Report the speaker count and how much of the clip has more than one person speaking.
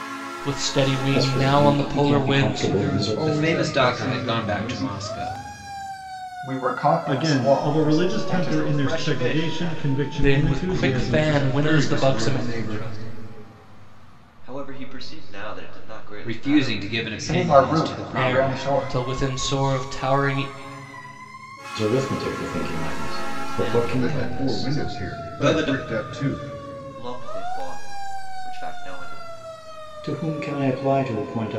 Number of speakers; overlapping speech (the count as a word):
seven, about 48%